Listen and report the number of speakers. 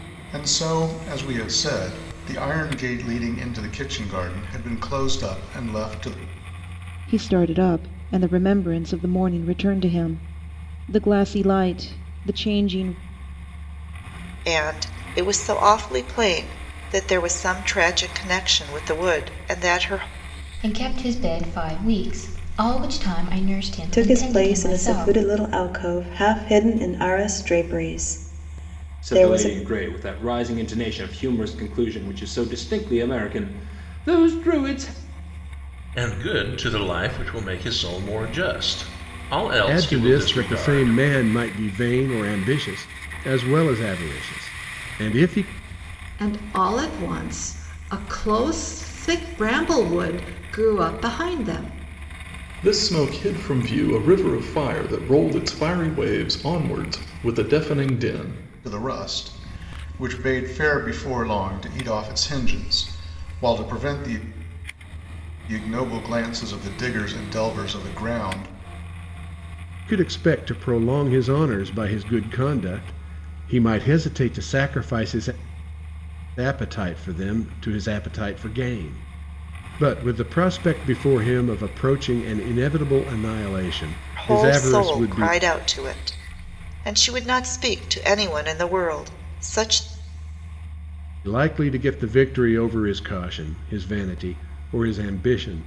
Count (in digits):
10